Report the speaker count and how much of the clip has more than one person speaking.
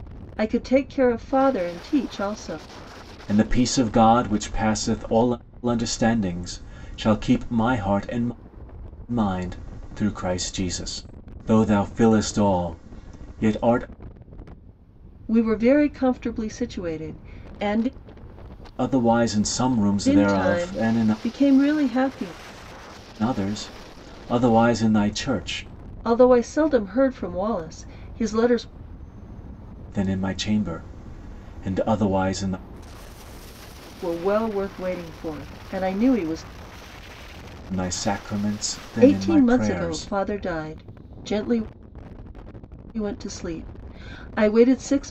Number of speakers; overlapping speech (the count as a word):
two, about 5%